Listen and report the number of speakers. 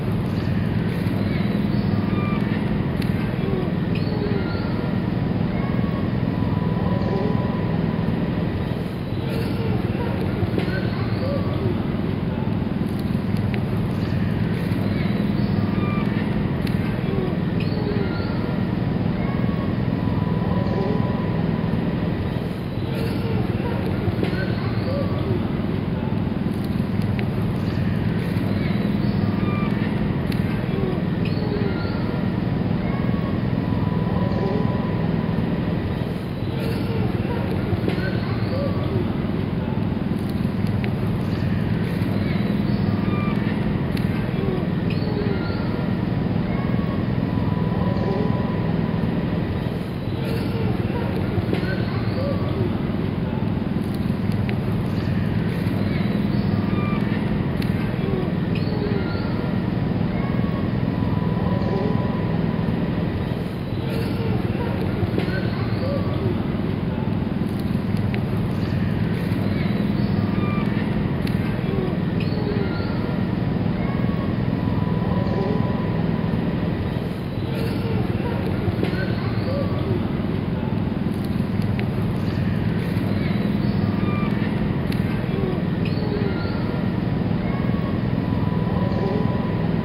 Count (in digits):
0